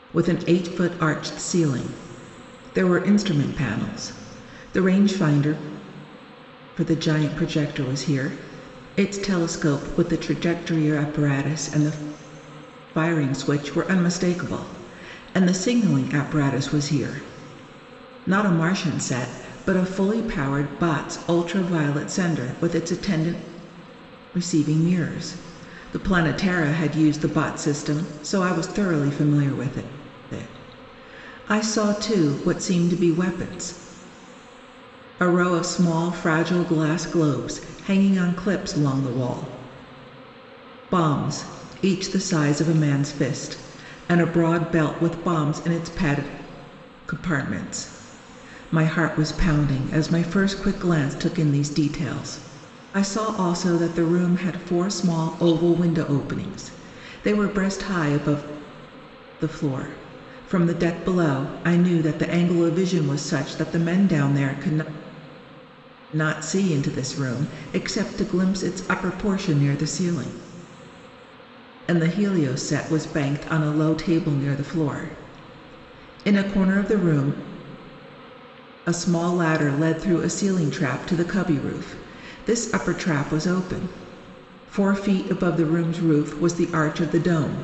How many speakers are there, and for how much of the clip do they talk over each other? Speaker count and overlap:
1, no overlap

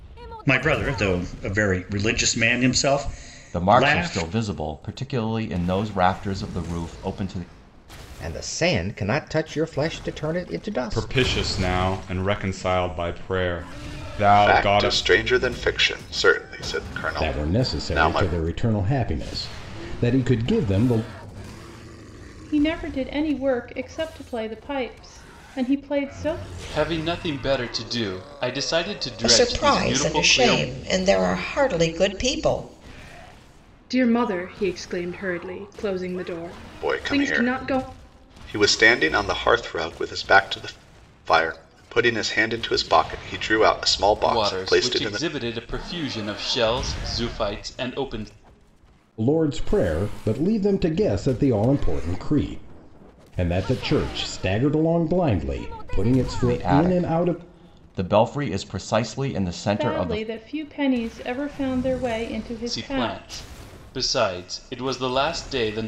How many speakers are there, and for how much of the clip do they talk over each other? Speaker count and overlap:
10, about 14%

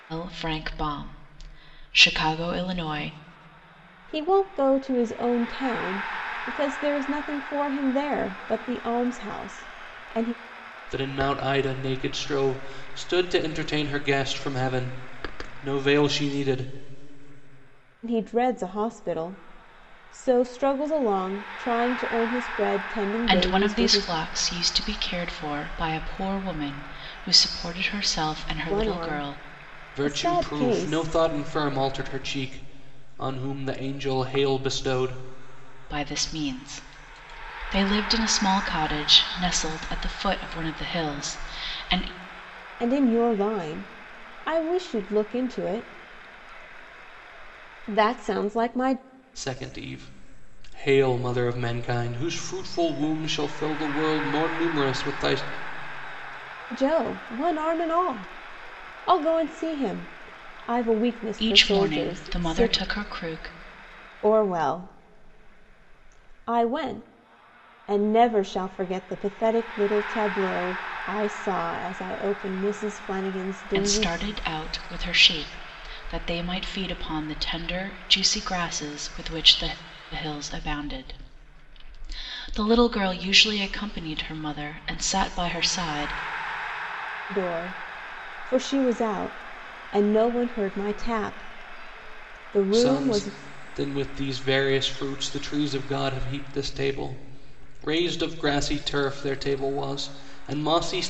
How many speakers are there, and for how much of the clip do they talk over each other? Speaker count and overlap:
3, about 5%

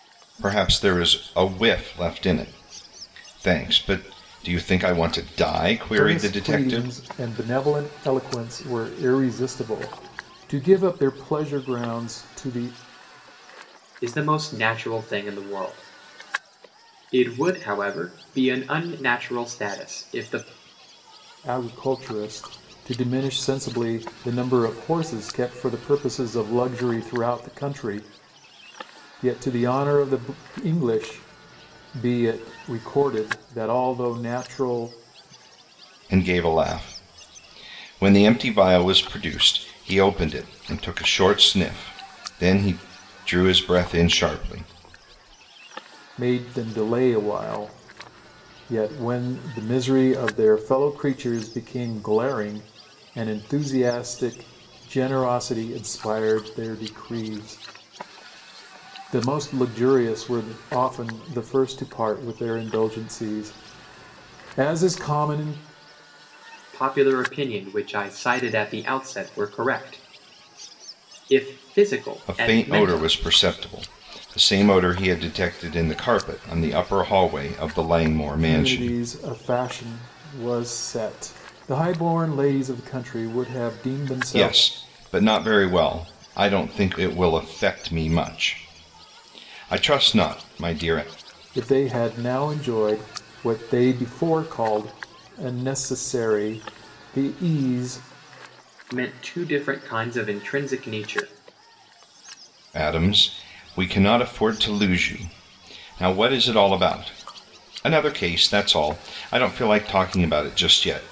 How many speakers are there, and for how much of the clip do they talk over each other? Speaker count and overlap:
3, about 3%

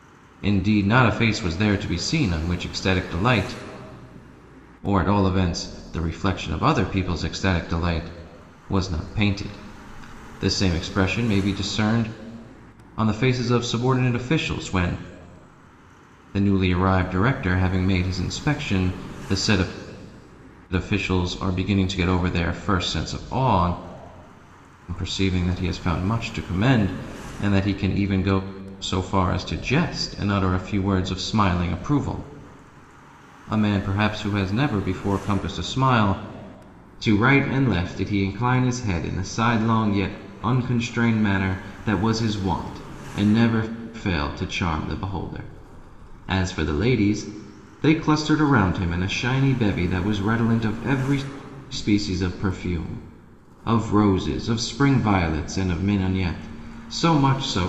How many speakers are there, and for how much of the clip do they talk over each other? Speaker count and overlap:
1, no overlap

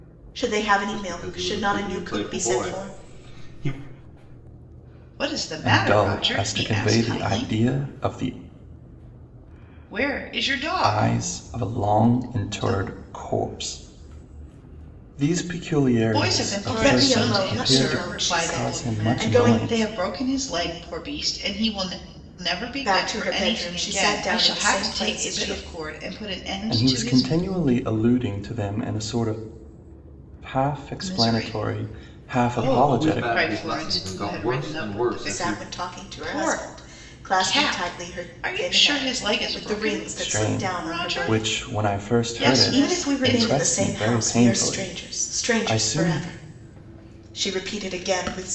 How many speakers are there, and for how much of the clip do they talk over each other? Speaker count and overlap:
4, about 57%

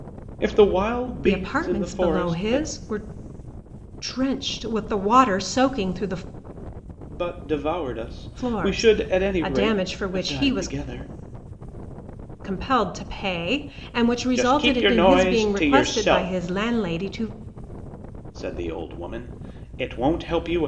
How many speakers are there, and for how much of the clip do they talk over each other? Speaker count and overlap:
2, about 30%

